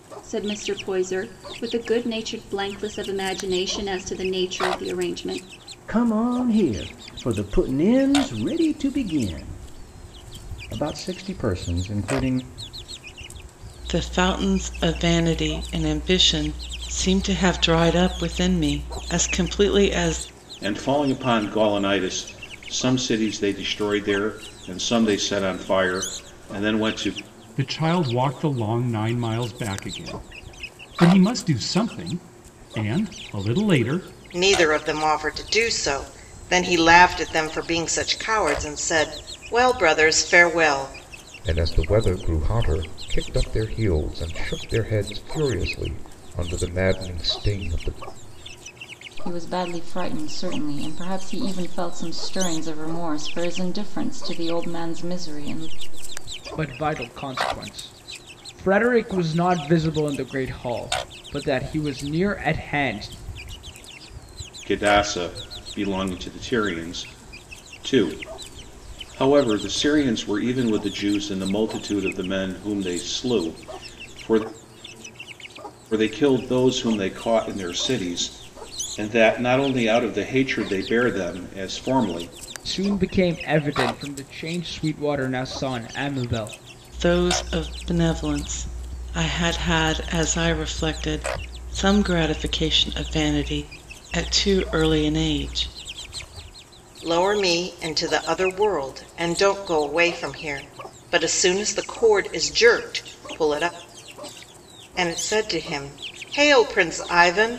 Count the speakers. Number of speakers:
nine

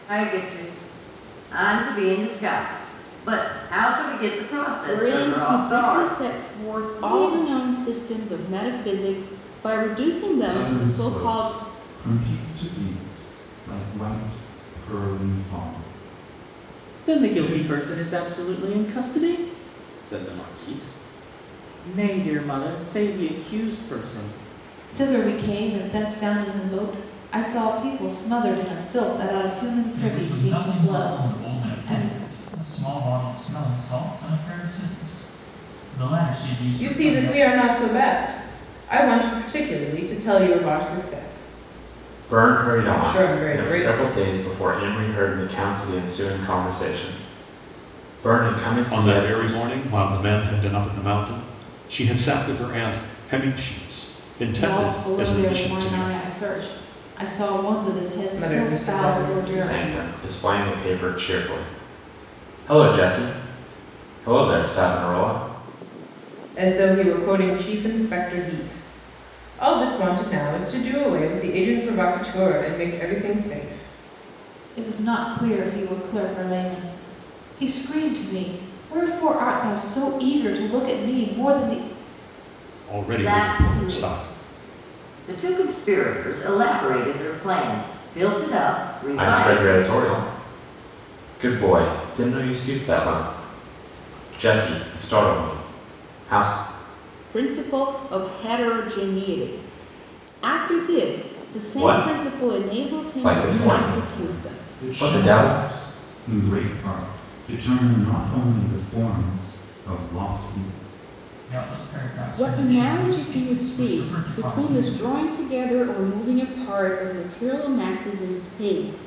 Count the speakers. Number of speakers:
nine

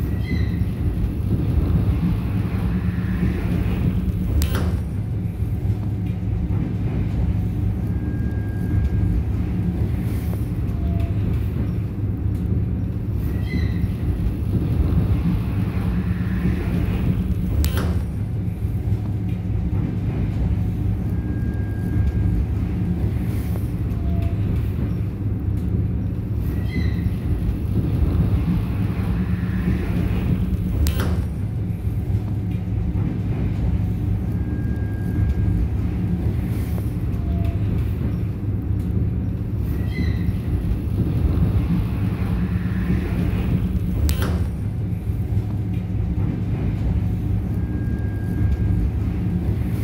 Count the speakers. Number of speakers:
zero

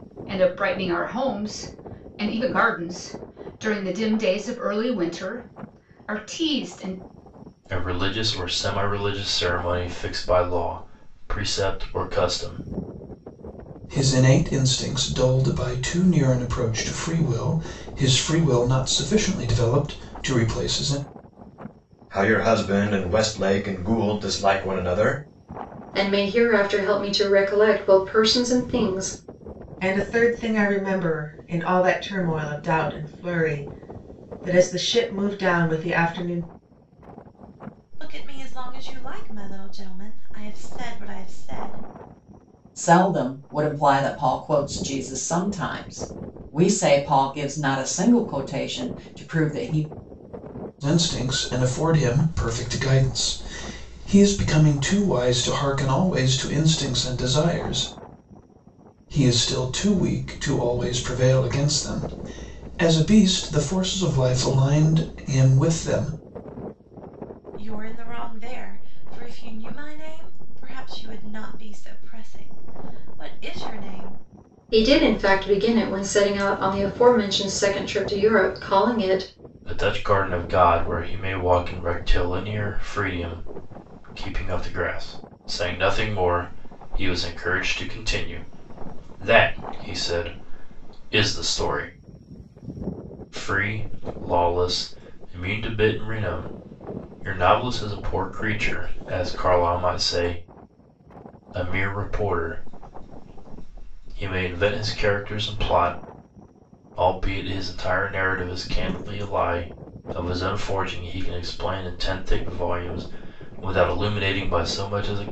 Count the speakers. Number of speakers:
eight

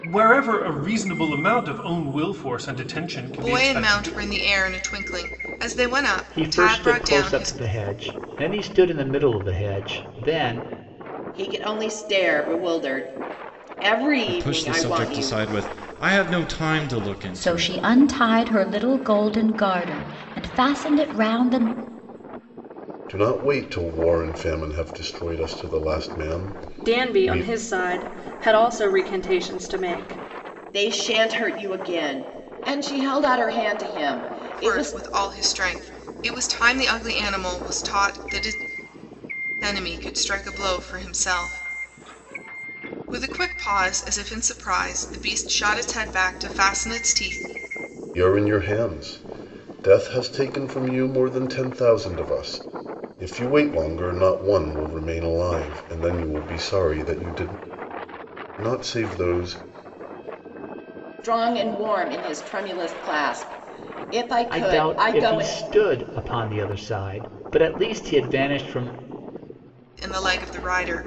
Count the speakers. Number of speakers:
eight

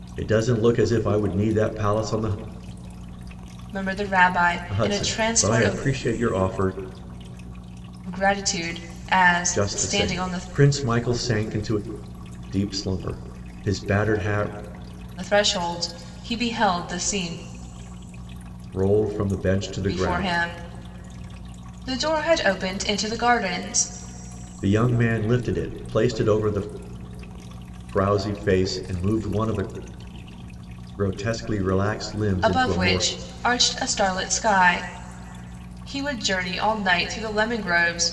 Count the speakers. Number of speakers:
two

